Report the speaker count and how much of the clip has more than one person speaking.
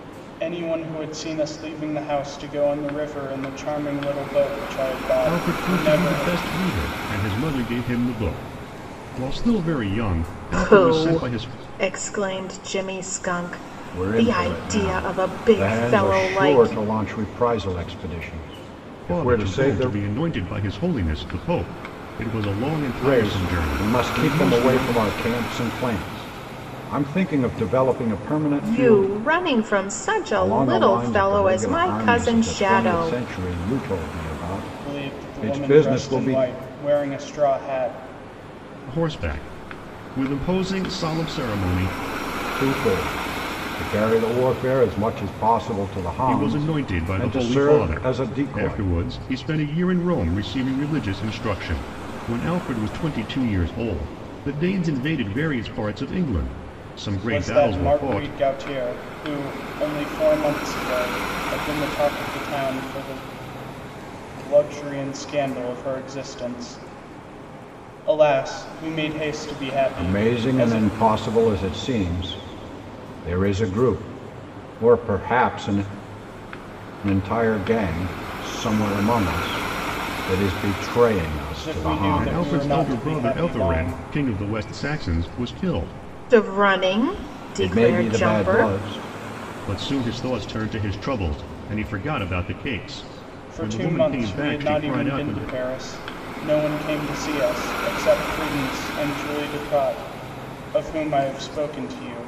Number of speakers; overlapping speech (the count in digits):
4, about 23%